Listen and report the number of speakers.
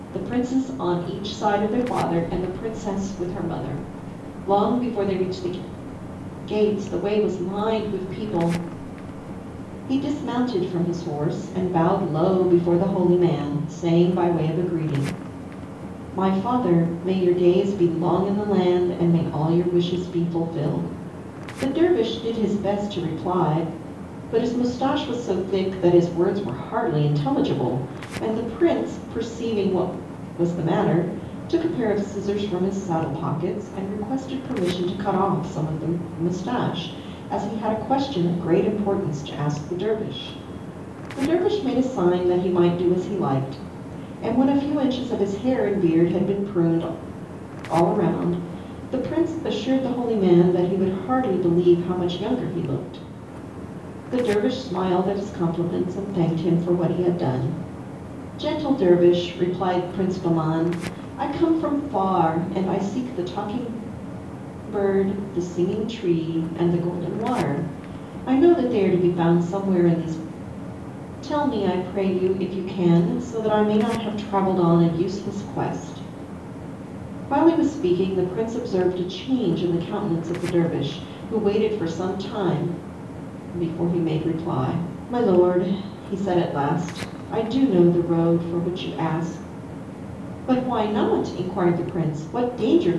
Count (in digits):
1